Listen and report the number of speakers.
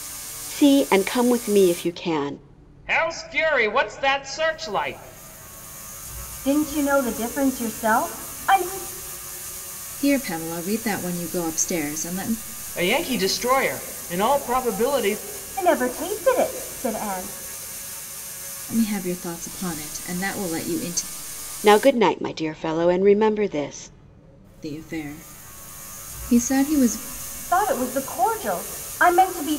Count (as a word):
four